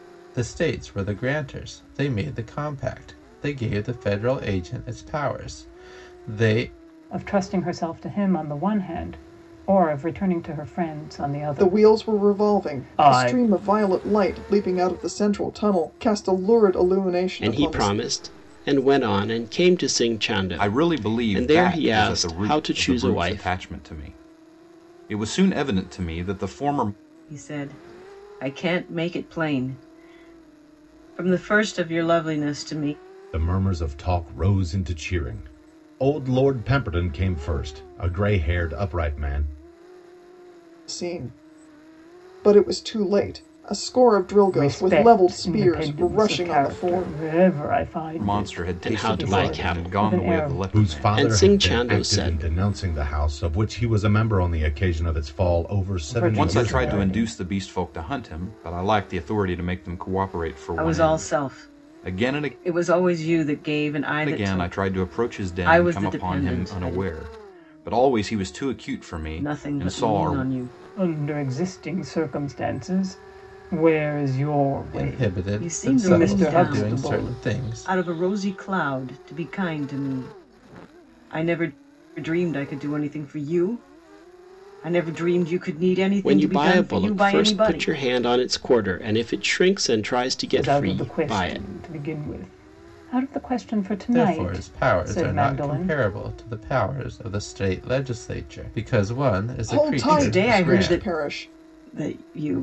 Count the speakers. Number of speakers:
7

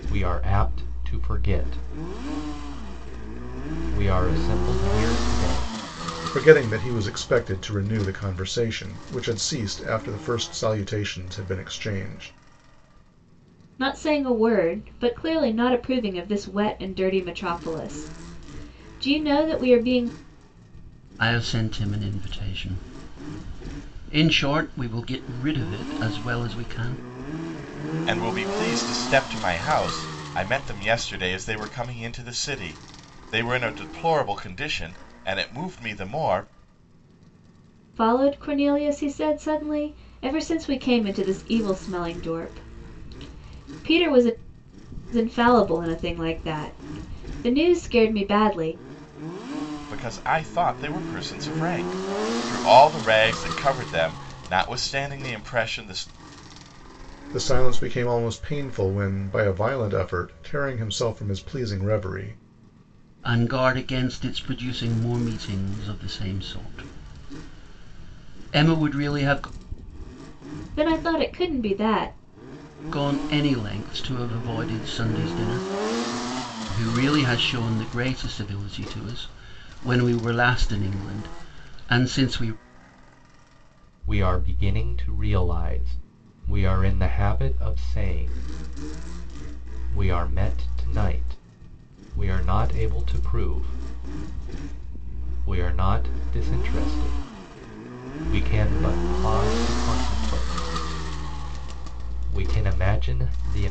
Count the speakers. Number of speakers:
5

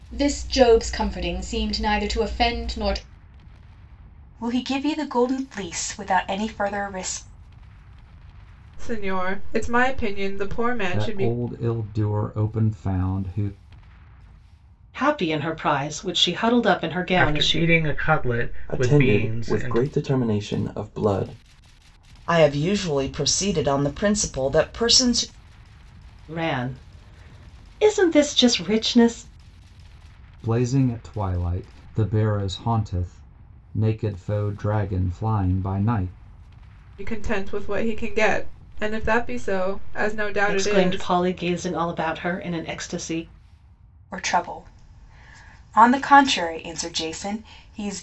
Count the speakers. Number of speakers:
8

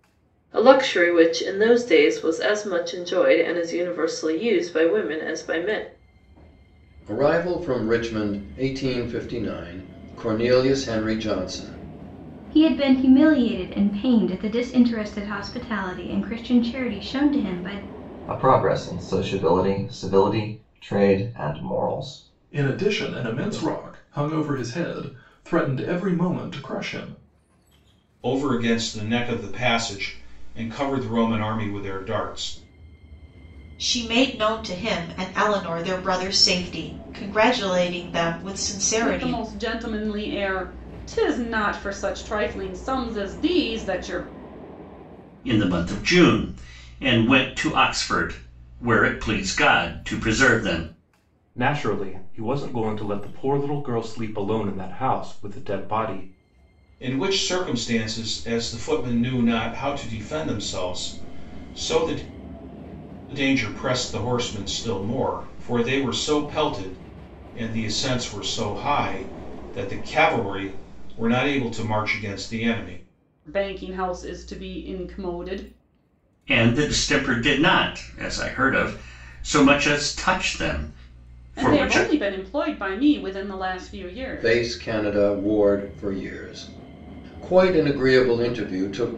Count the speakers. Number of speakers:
10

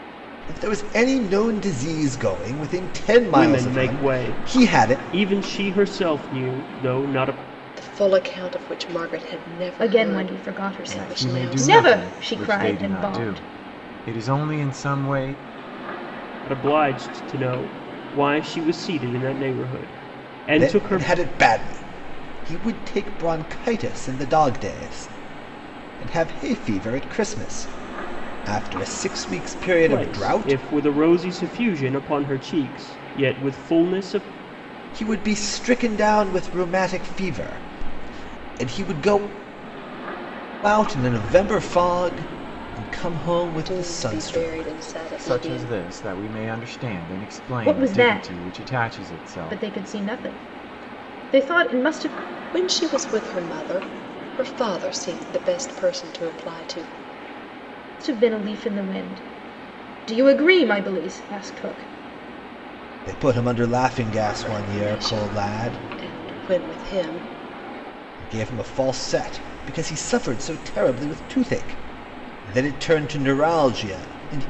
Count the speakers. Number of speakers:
5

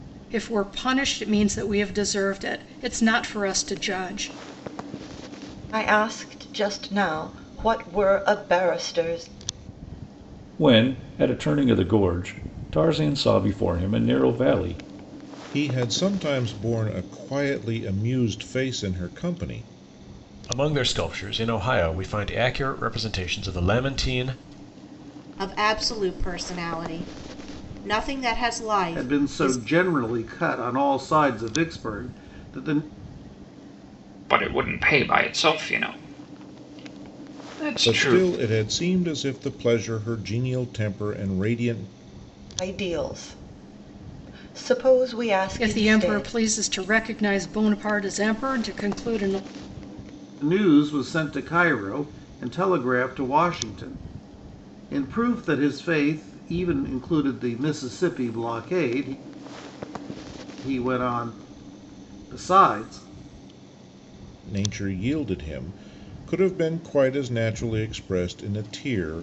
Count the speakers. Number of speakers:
8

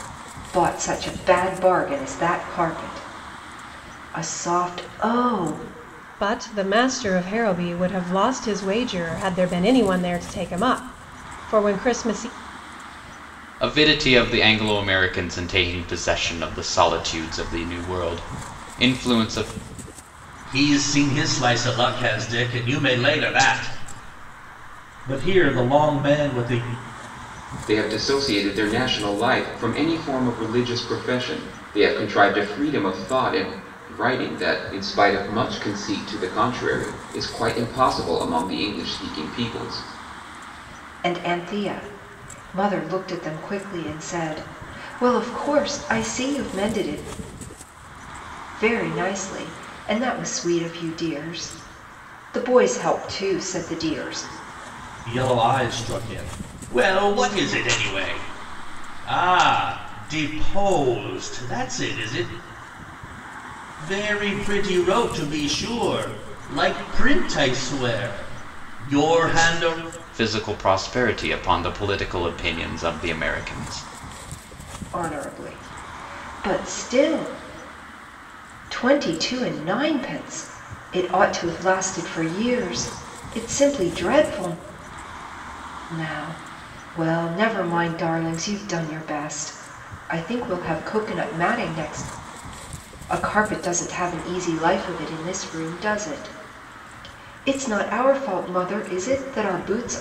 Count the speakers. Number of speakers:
5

